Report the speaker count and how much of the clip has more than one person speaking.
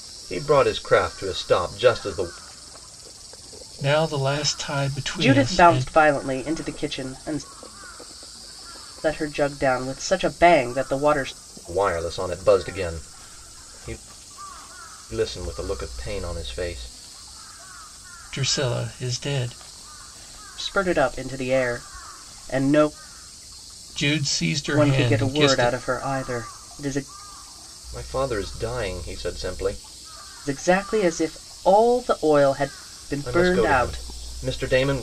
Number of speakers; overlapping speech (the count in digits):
3, about 8%